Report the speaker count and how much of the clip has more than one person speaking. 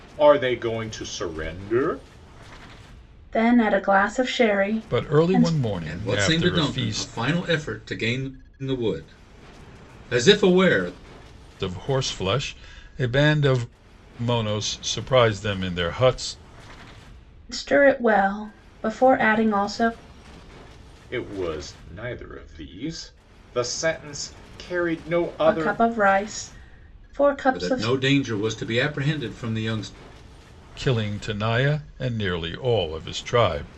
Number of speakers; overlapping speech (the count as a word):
four, about 8%